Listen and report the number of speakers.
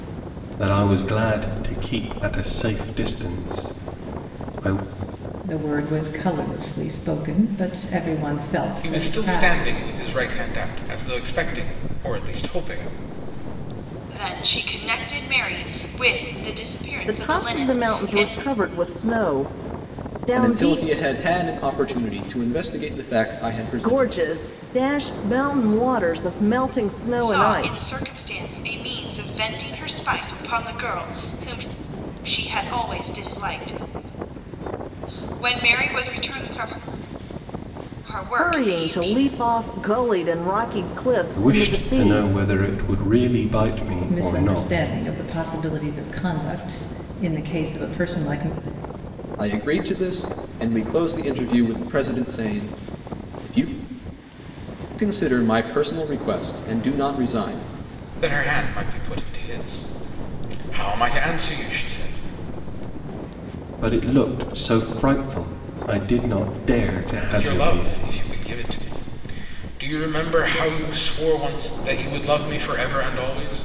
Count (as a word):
six